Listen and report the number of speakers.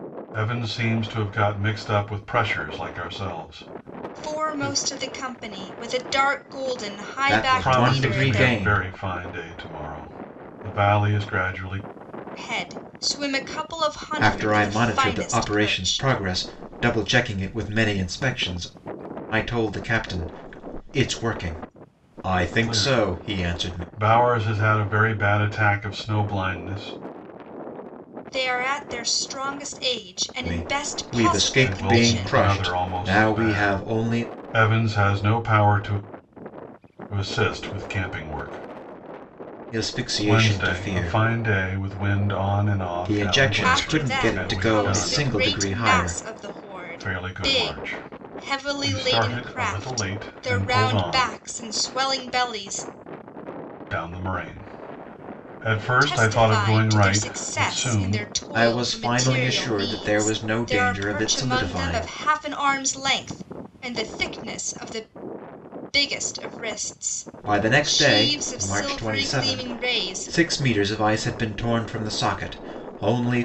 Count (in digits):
3